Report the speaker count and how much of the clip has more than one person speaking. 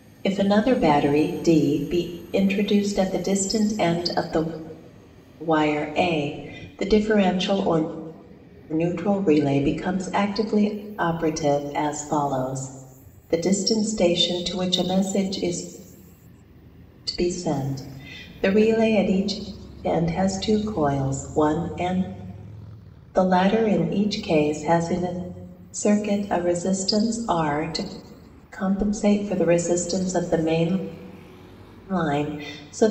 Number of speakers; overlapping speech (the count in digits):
1, no overlap